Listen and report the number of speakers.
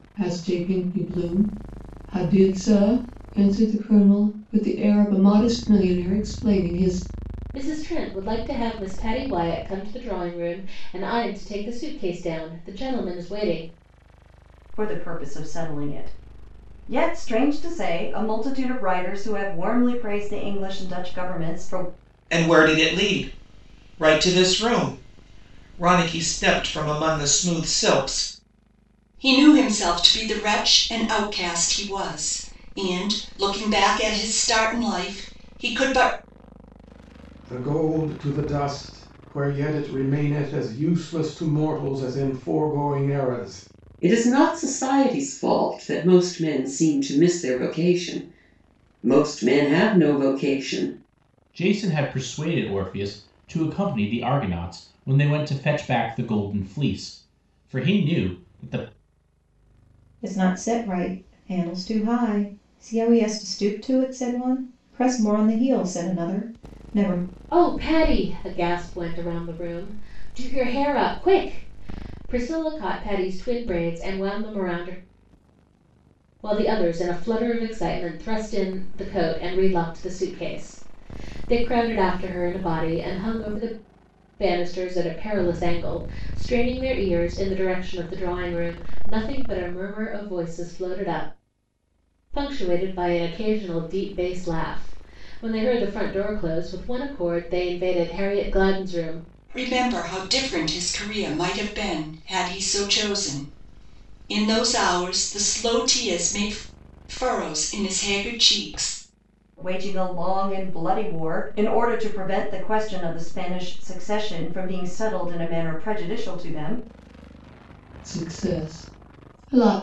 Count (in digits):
9